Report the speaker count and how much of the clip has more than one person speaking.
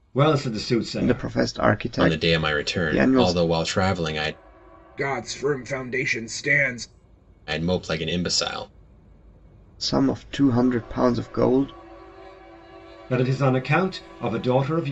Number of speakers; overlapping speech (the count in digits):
4, about 12%